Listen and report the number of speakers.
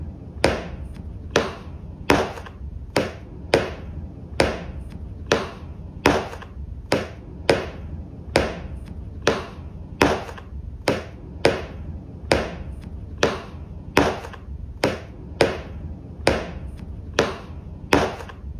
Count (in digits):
0